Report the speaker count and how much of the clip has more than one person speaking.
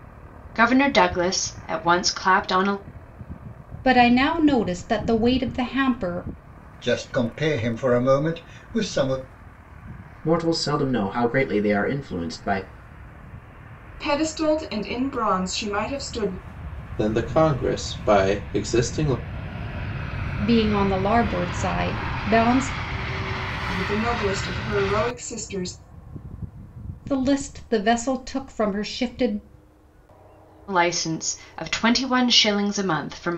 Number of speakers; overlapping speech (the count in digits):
6, no overlap